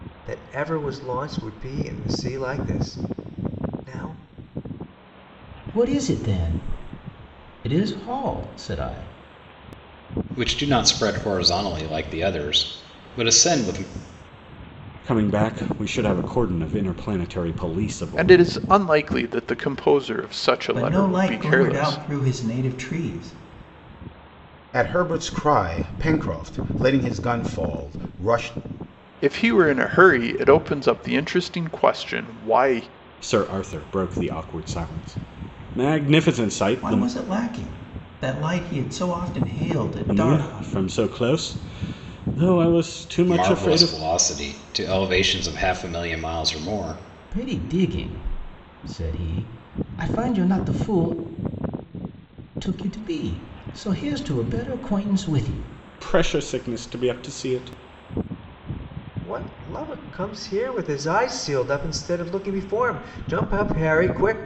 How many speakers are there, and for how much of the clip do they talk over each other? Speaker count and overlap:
seven, about 5%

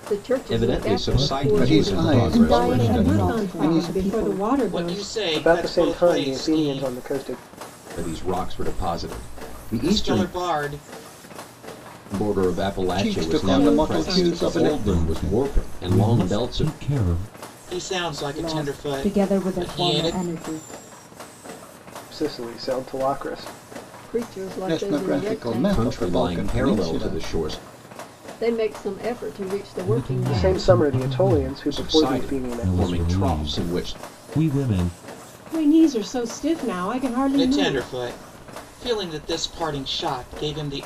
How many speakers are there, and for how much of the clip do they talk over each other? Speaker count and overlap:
eight, about 48%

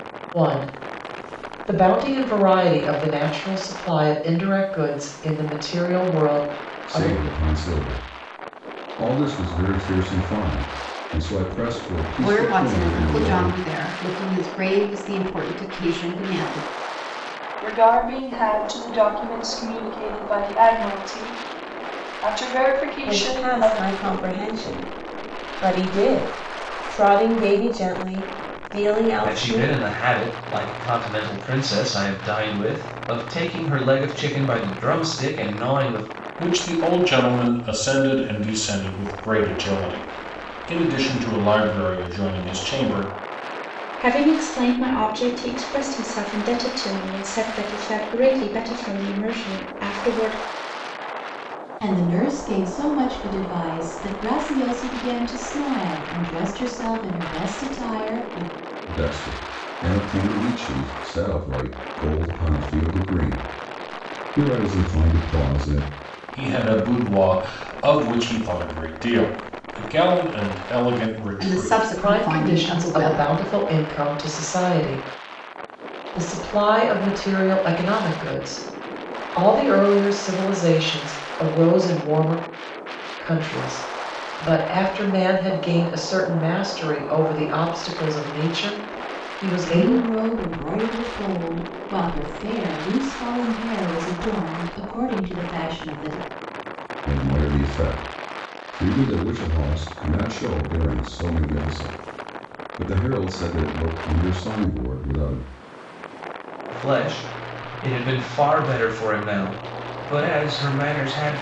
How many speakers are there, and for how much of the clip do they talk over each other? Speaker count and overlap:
nine, about 5%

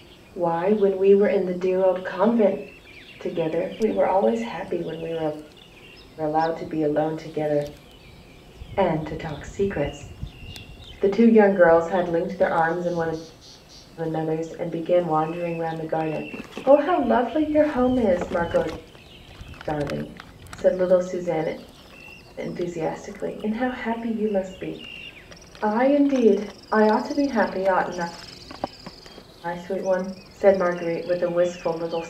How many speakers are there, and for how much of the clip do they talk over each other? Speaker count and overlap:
one, no overlap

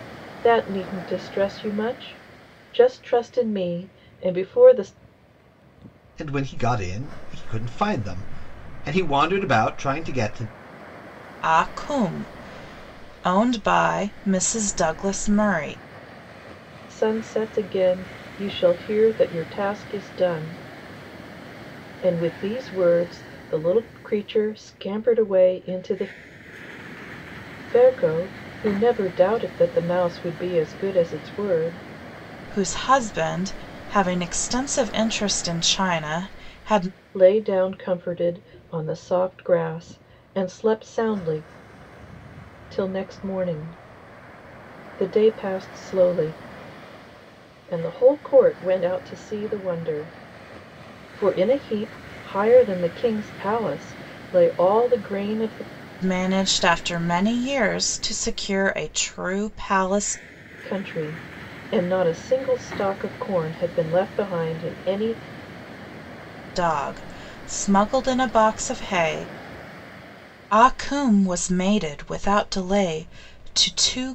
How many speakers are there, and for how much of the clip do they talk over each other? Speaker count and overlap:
three, no overlap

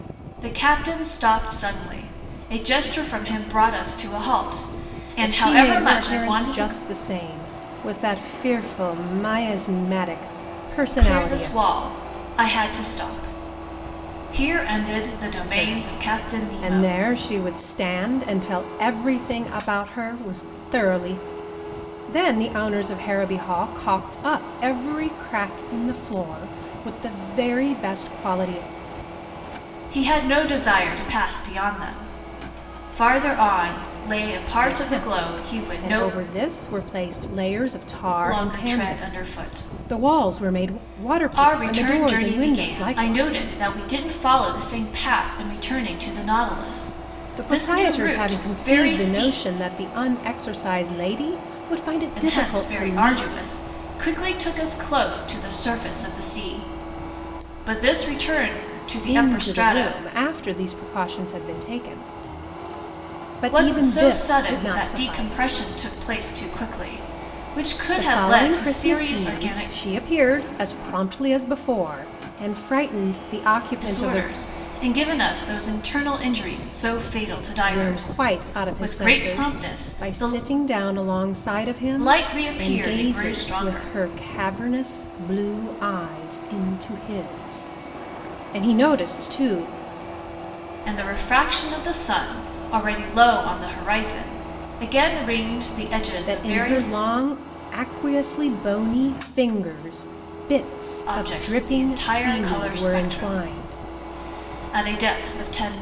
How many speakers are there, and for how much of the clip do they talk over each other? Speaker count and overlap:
two, about 26%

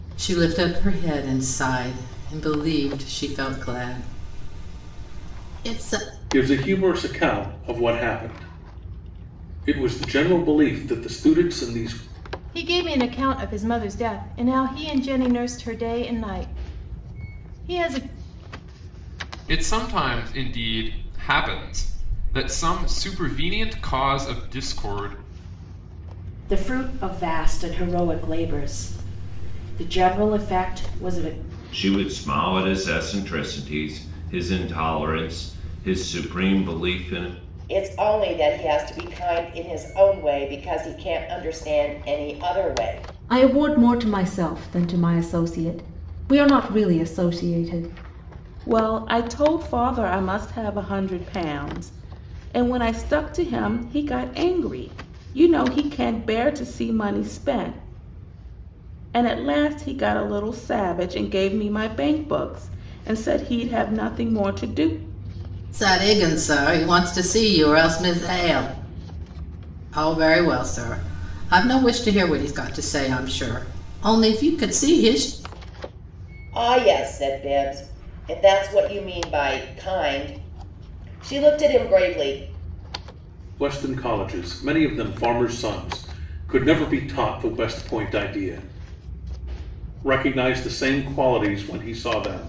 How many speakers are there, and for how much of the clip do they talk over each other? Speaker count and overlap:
nine, no overlap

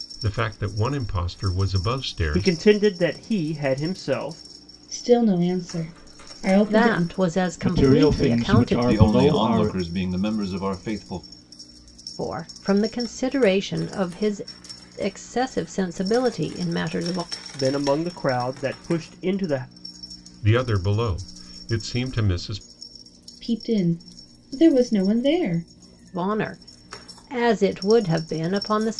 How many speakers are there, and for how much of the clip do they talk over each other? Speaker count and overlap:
six, about 10%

